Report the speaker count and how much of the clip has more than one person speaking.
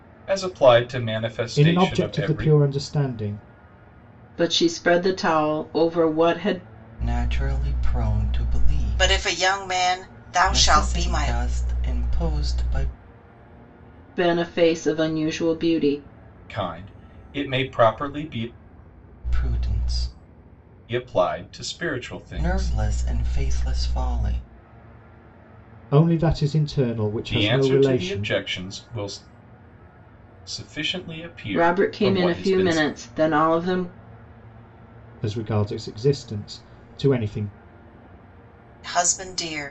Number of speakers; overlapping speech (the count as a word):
five, about 13%